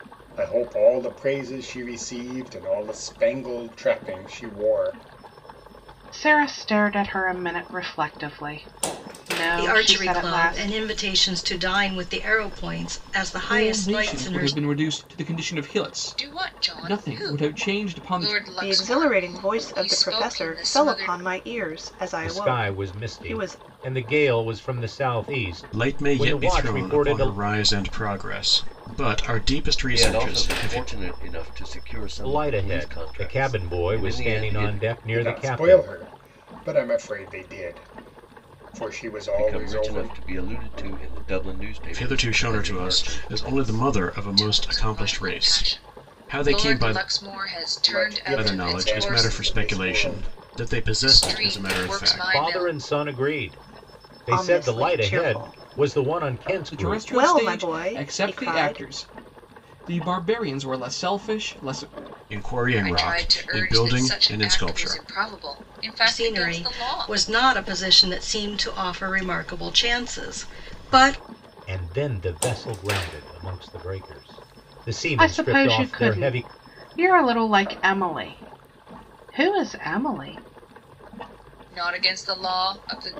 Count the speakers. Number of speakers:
9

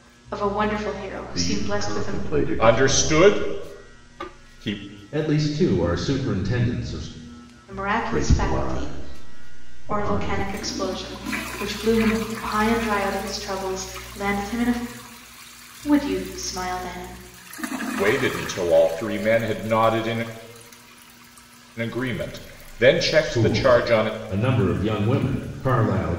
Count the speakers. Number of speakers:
4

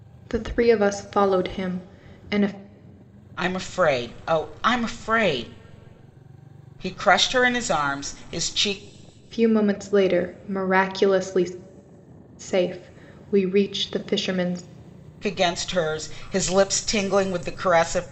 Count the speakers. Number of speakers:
2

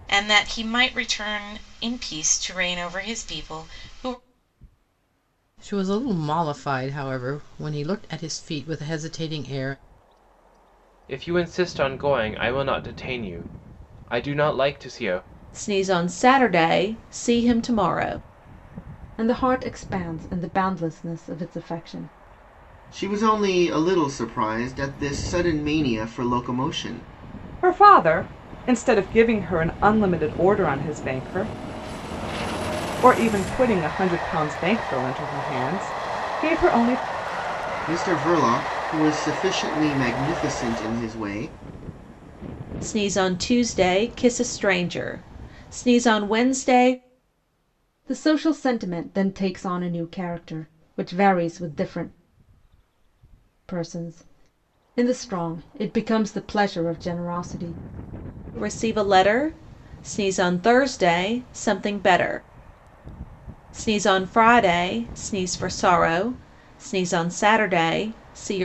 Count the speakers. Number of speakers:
7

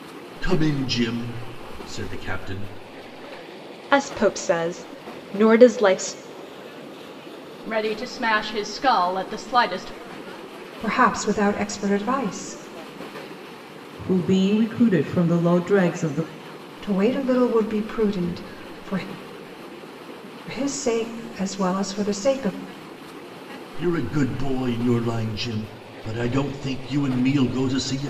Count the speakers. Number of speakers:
5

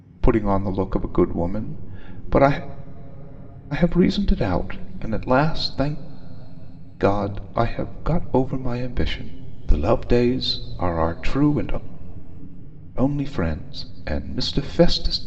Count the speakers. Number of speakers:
1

